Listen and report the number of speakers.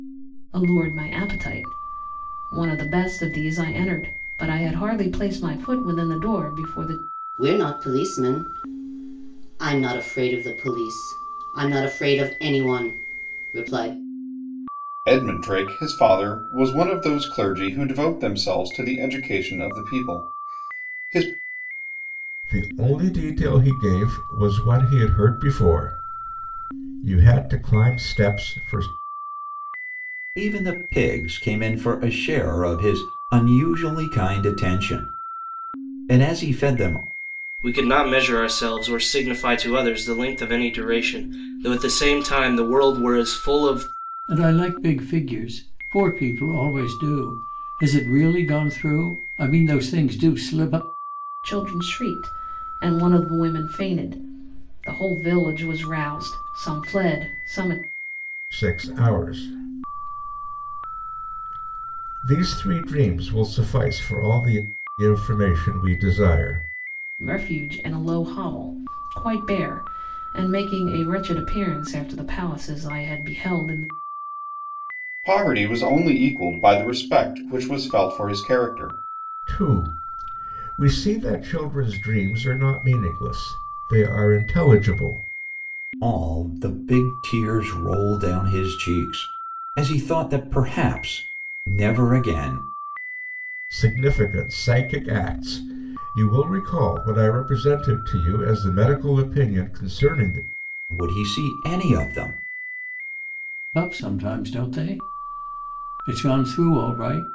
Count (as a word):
seven